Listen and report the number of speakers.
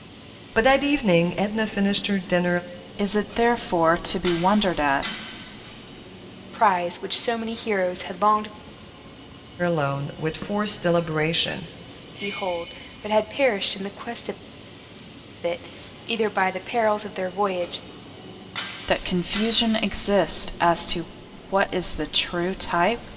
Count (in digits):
3